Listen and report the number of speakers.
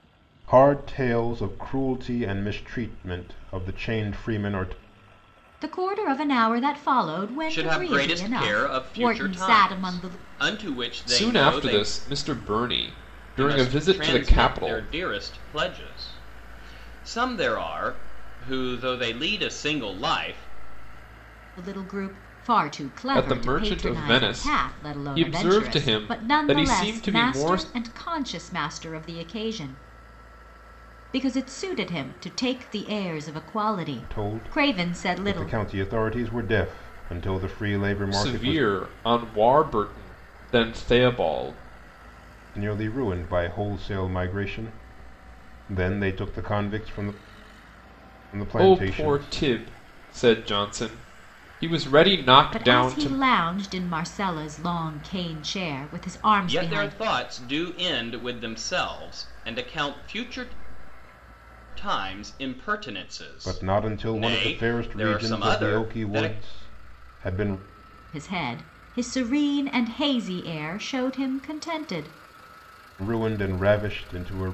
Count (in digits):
4